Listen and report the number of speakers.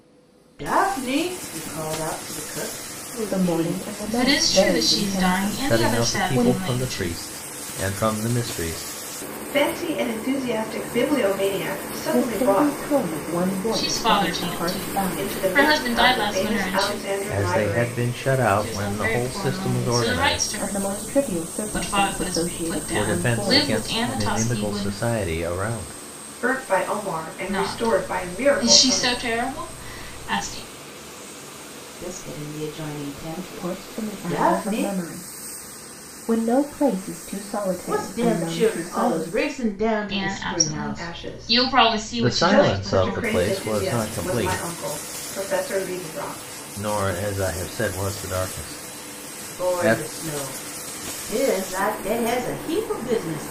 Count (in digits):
5